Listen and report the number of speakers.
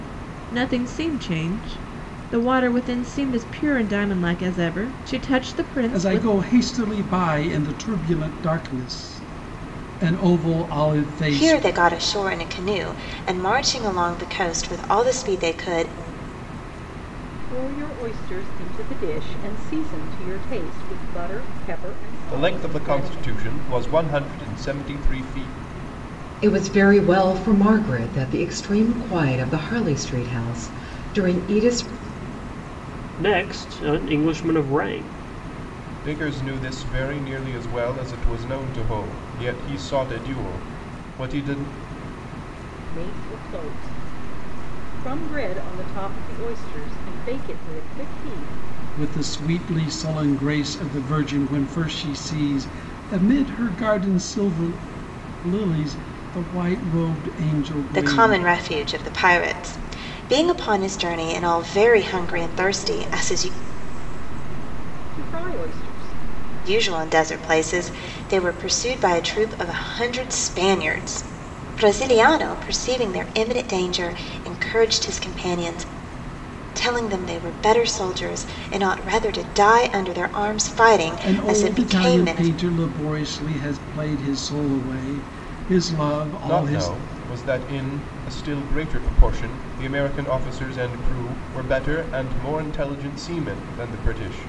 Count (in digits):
7